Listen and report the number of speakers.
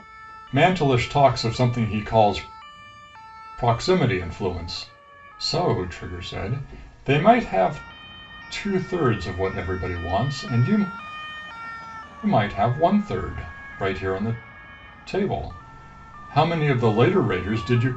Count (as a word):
one